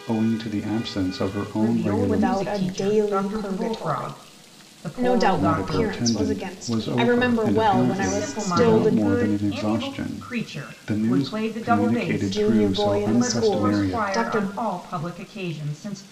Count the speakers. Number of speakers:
3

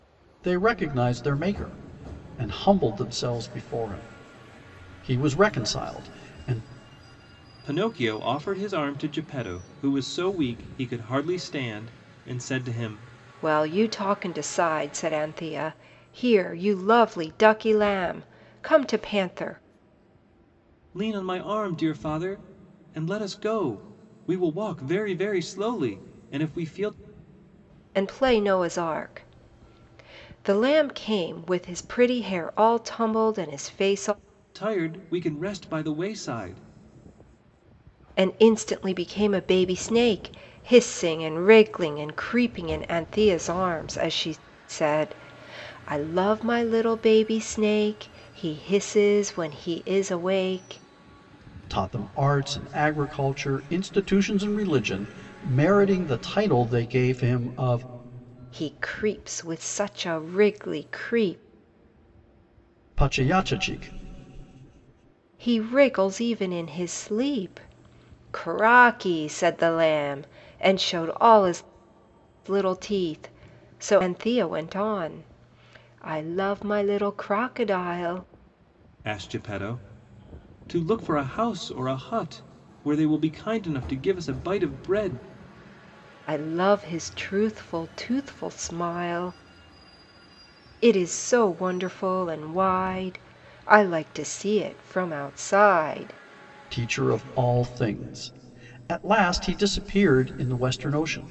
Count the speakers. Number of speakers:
3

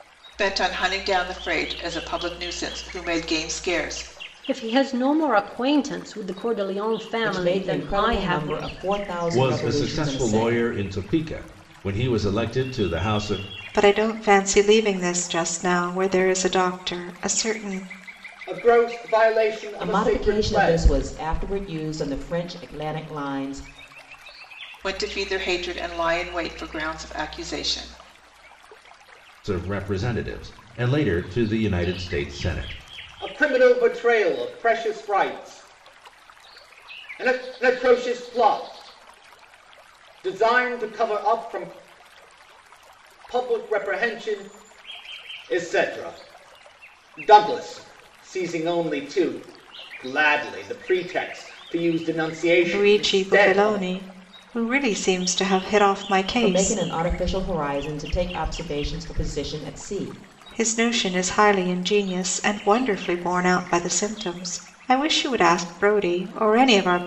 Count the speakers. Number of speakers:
6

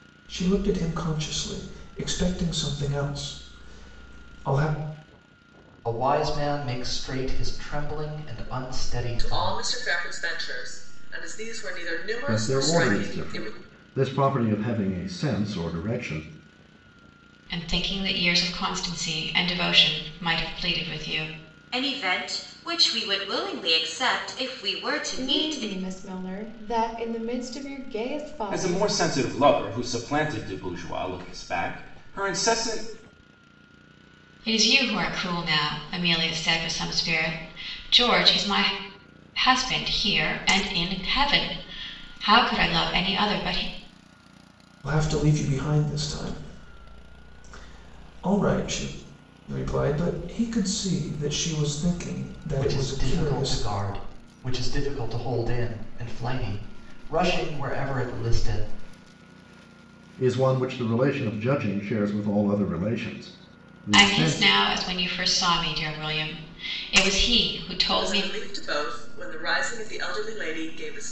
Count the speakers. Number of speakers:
8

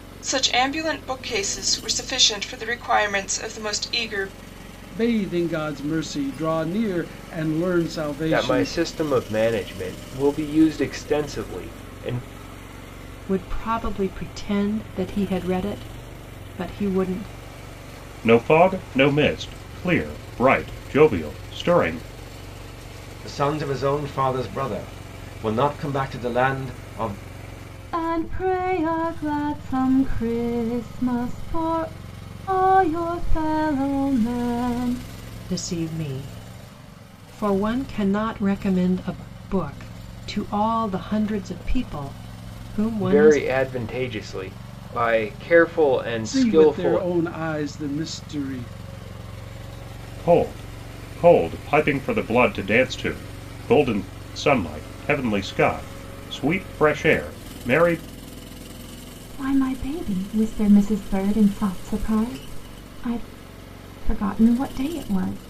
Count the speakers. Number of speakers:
7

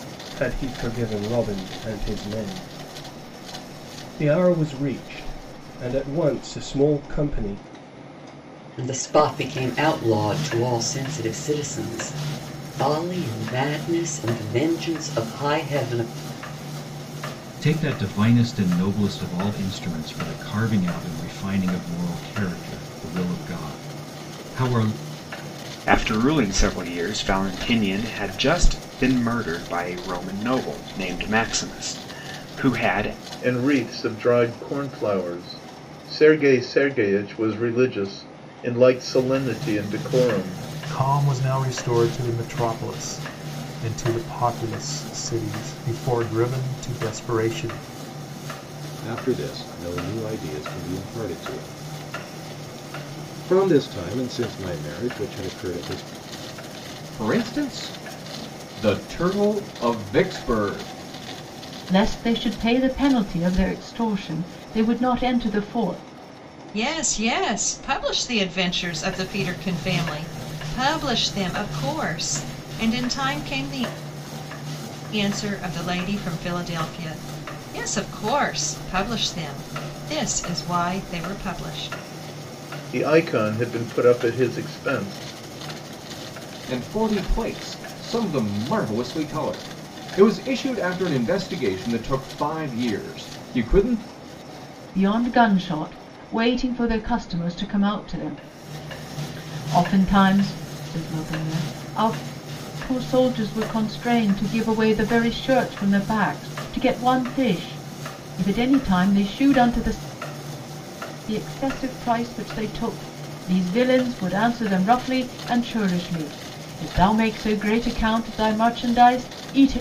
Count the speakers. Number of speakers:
10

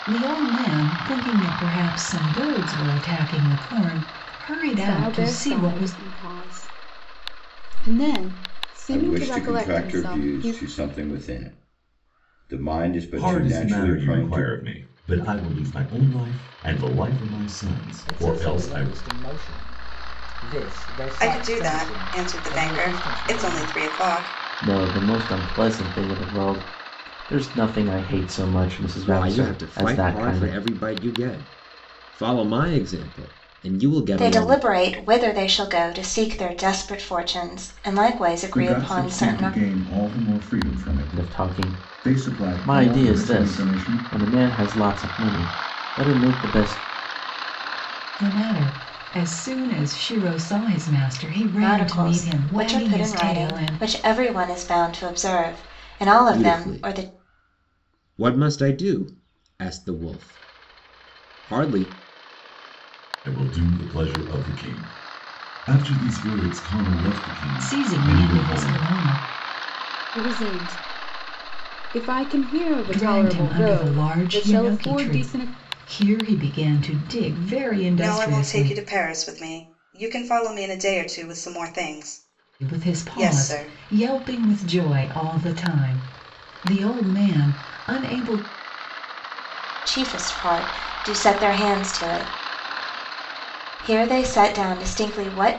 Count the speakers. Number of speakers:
10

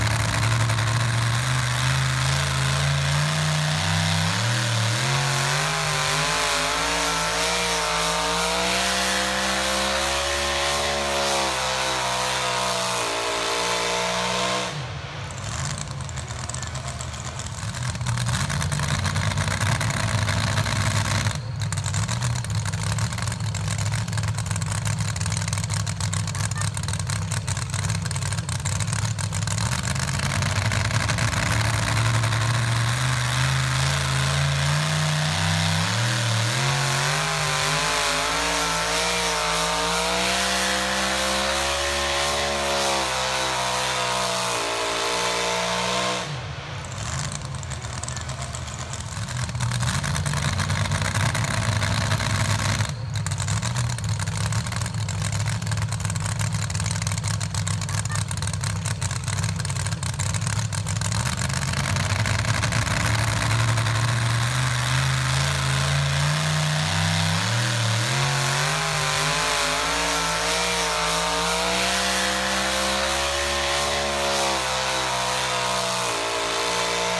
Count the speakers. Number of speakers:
0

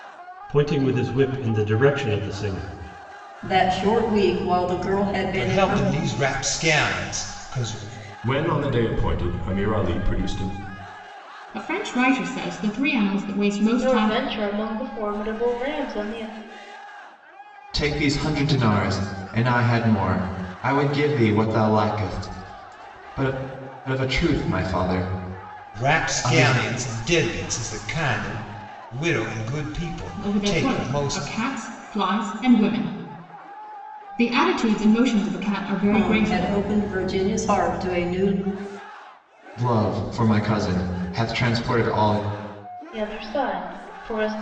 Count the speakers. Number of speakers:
7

